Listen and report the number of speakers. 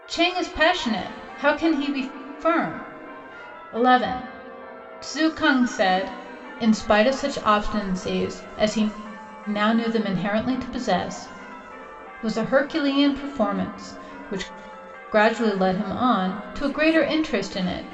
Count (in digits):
1